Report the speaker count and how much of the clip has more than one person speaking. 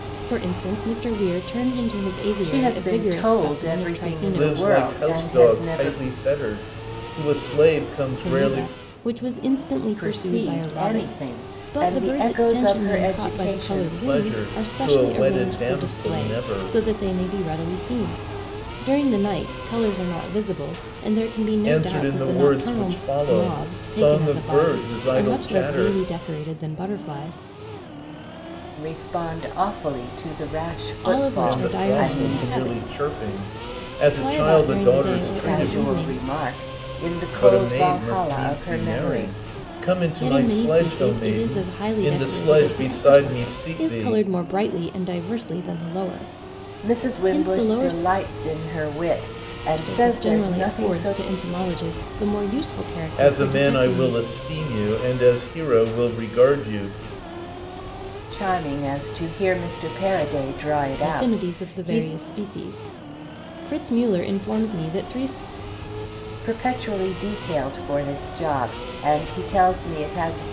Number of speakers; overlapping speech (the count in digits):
3, about 42%